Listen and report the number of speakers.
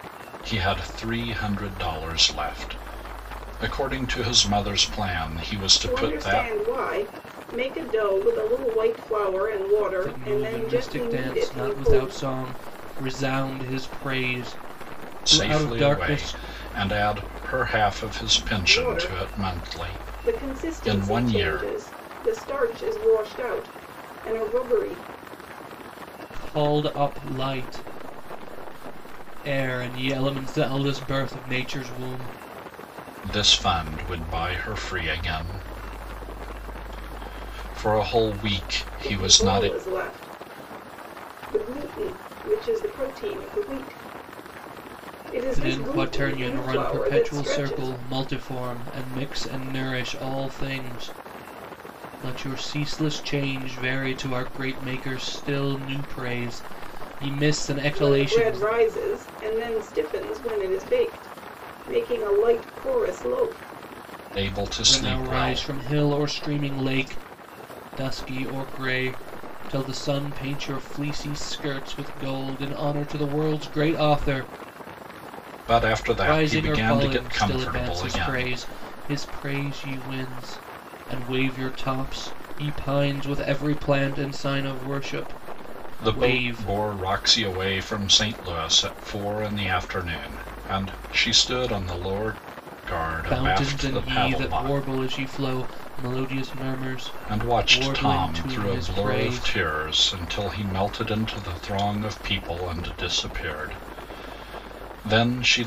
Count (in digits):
3